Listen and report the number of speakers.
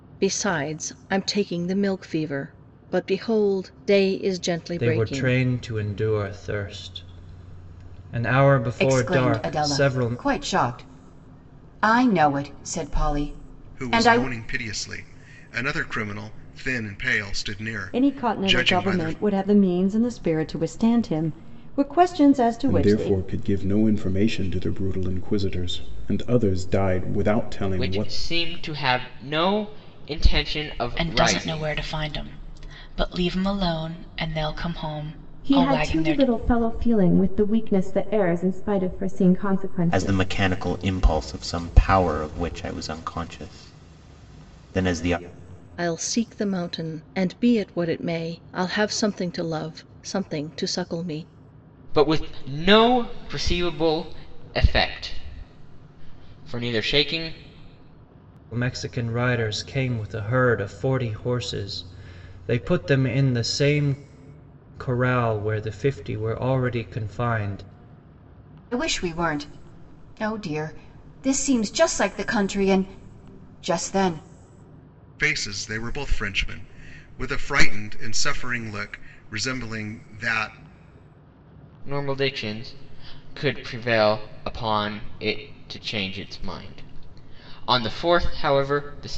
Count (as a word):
ten